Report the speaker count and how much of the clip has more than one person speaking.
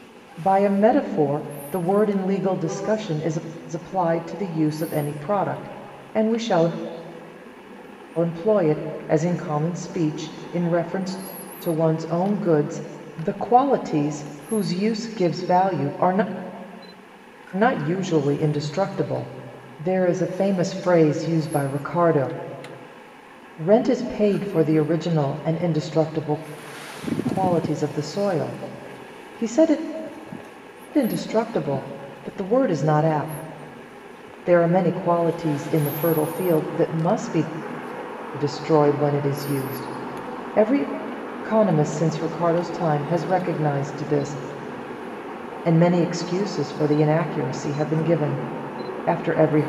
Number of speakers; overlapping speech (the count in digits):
1, no overlap